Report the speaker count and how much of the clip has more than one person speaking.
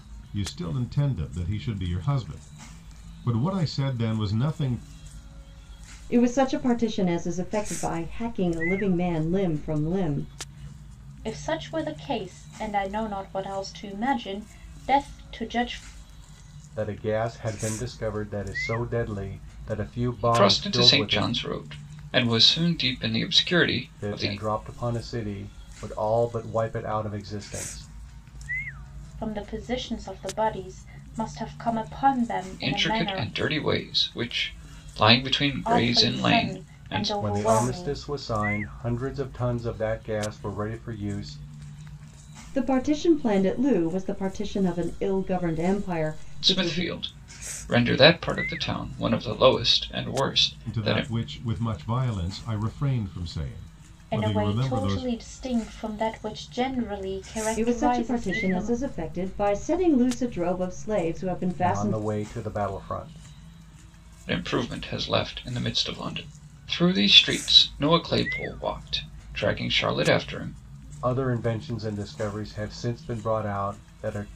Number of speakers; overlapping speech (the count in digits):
5, about 11%